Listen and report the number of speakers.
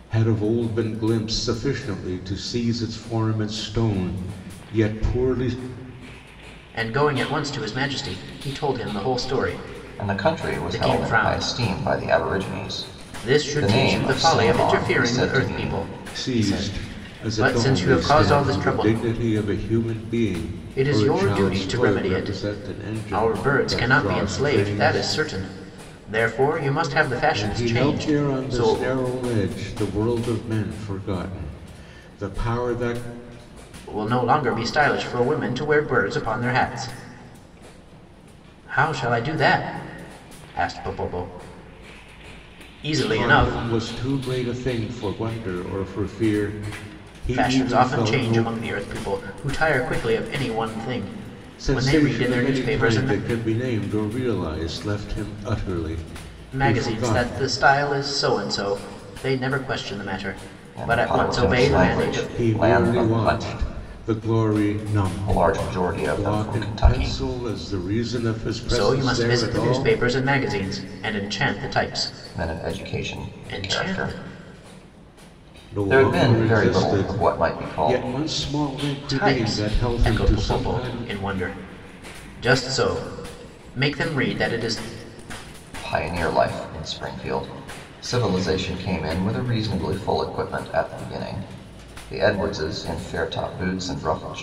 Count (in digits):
3